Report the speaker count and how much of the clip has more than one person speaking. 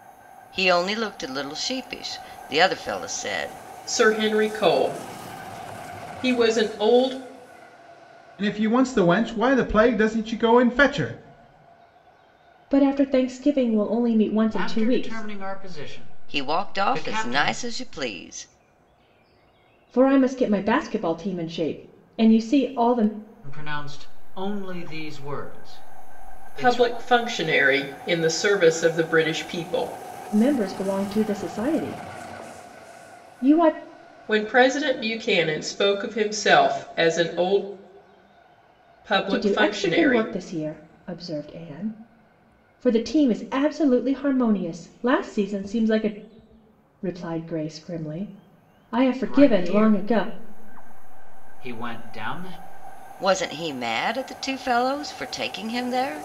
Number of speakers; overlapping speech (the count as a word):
five, about 8%